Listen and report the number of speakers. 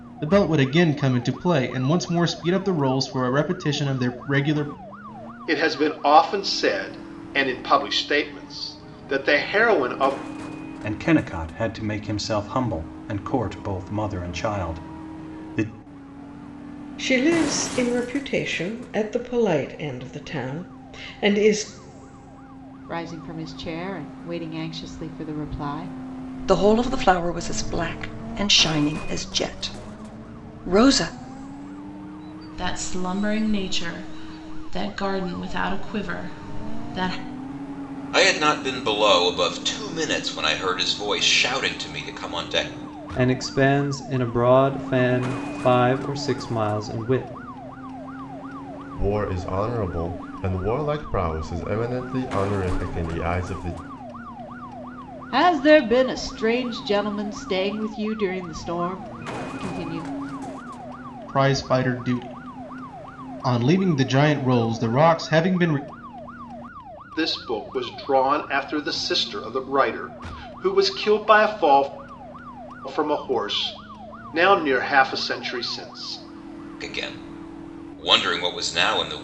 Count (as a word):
ten